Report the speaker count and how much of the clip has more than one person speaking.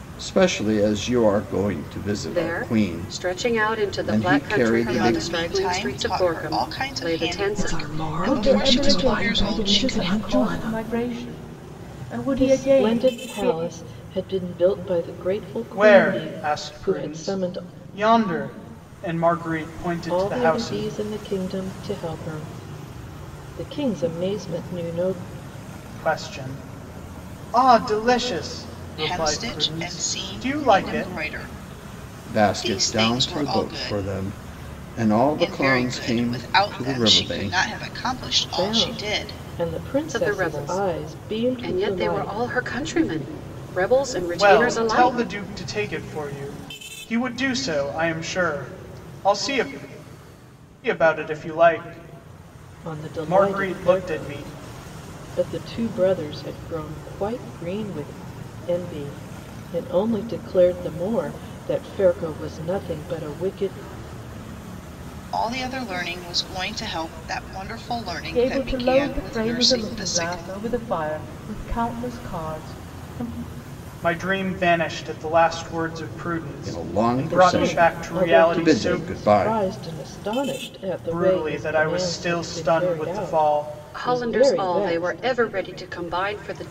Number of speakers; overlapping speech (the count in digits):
7, about 39%